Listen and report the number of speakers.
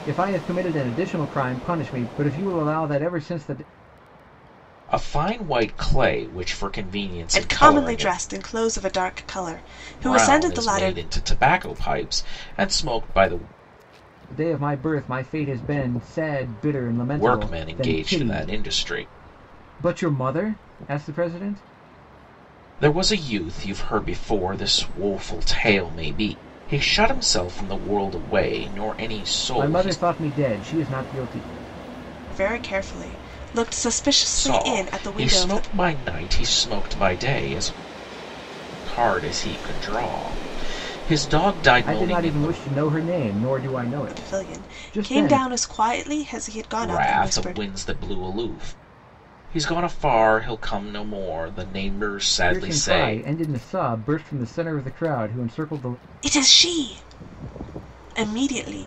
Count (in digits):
3